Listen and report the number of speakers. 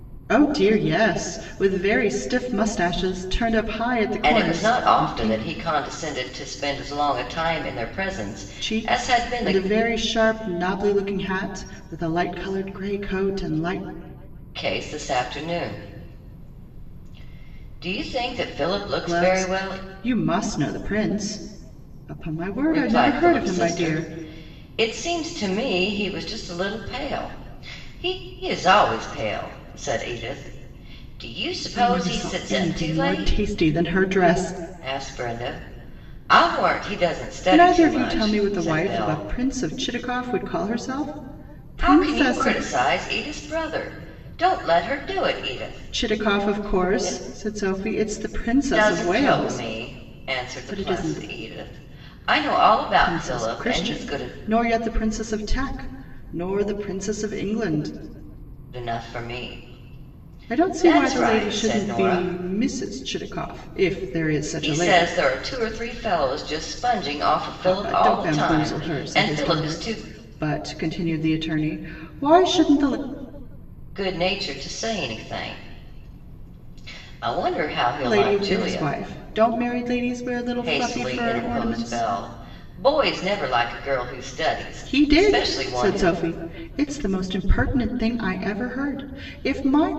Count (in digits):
2